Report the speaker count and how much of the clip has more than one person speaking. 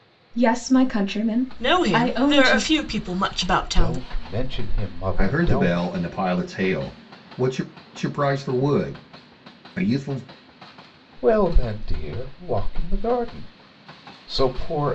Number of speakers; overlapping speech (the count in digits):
4, about 14%